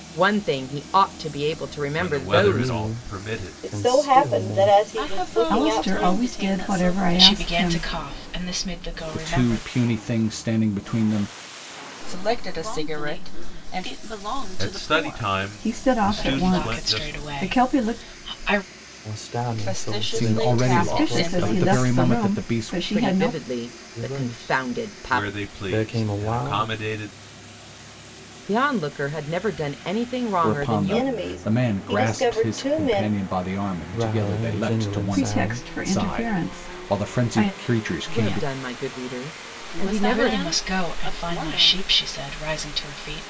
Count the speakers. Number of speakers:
9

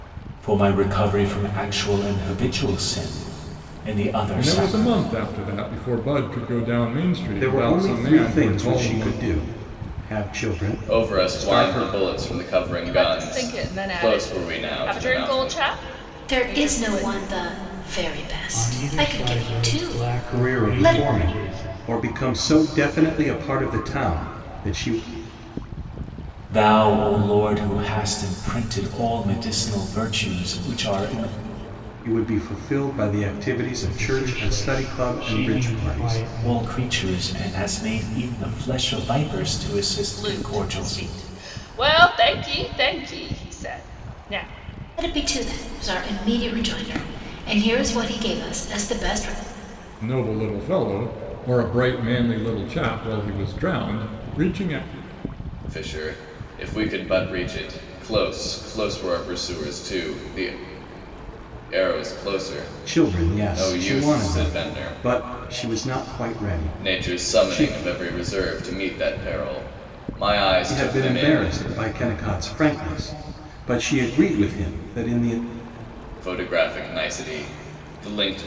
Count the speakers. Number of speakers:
7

